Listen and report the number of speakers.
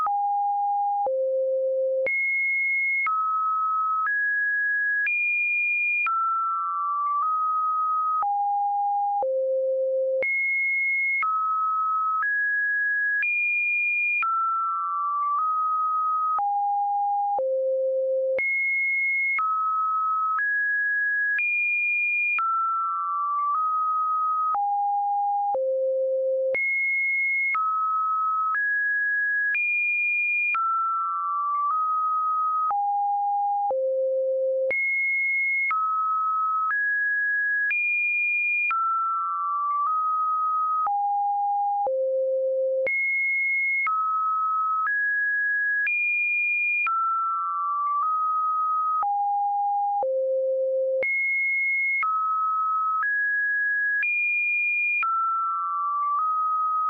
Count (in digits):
0